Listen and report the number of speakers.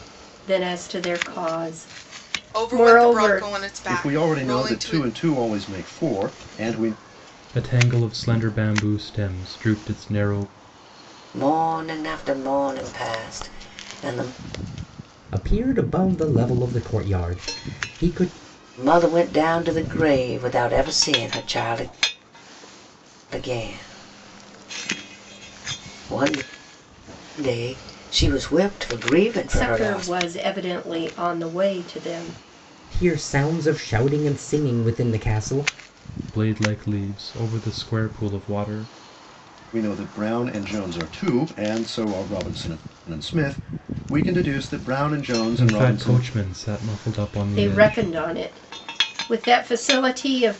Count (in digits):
6